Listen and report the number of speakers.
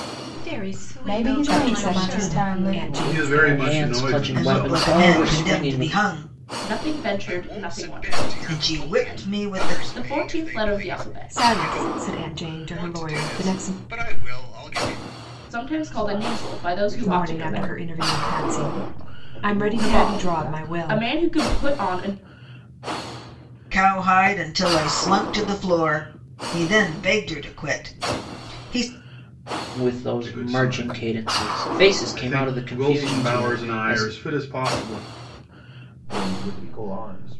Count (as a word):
nine